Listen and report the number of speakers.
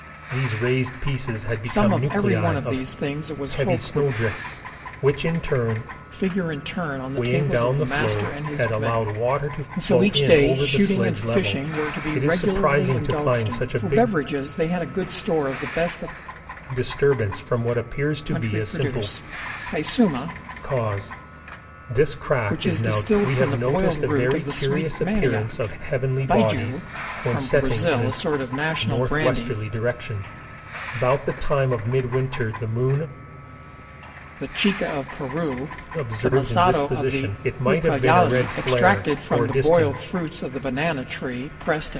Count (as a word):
two